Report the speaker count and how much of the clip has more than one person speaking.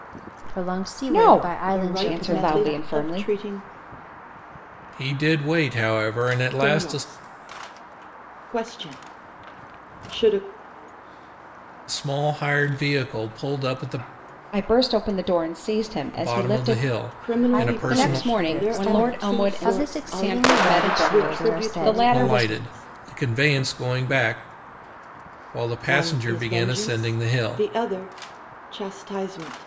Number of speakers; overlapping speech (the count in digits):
4, about 37%